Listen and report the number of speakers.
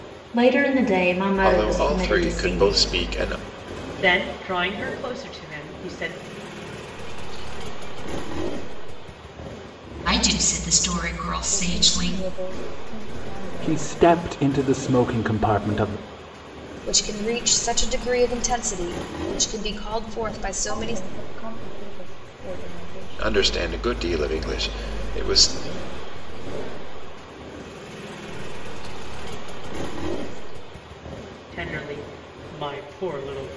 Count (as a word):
eight